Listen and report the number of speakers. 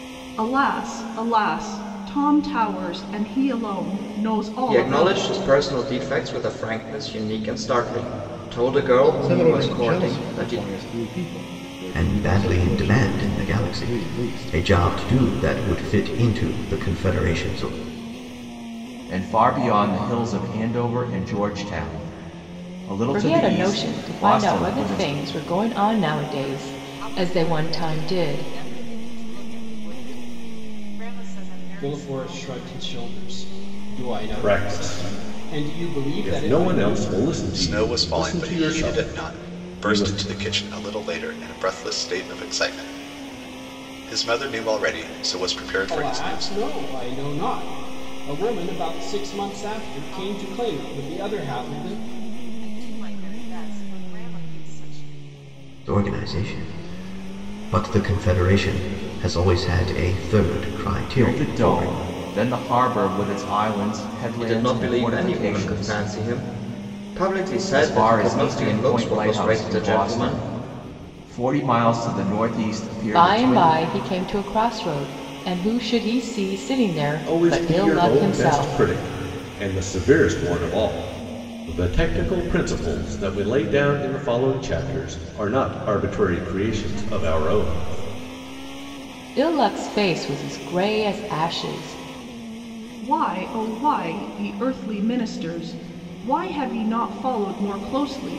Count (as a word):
ten